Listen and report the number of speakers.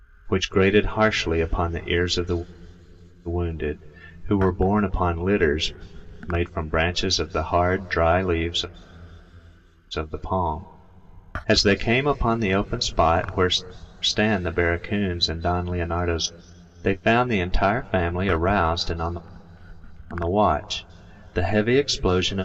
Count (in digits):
1